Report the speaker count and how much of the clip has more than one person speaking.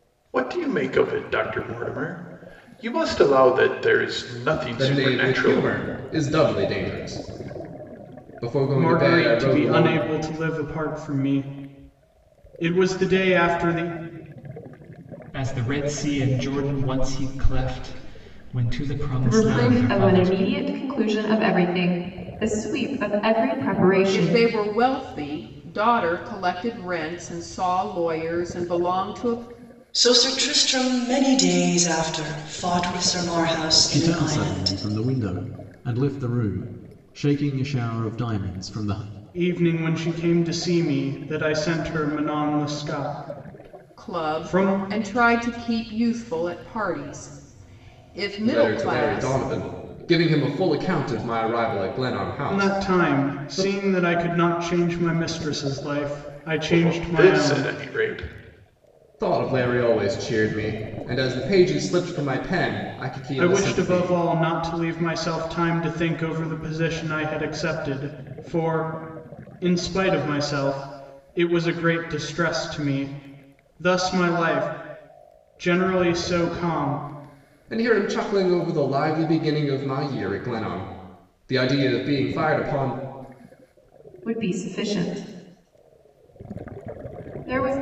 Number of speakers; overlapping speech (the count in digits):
8, about 11%